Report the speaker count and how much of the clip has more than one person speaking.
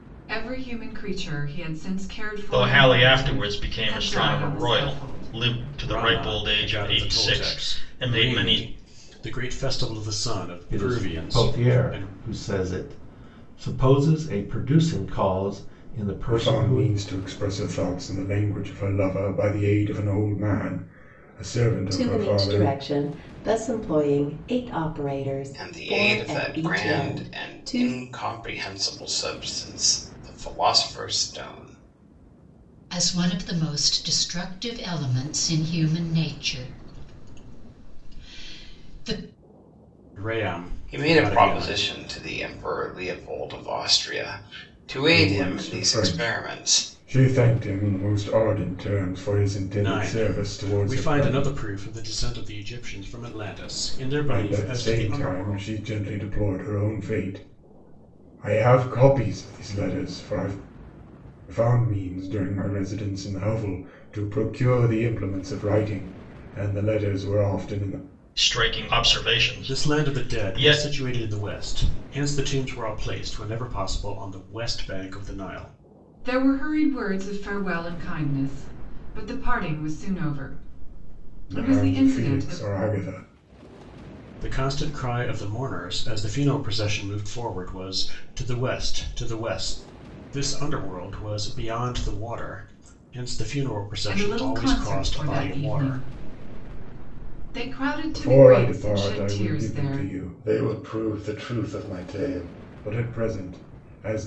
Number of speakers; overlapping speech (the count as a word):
eight, about 23%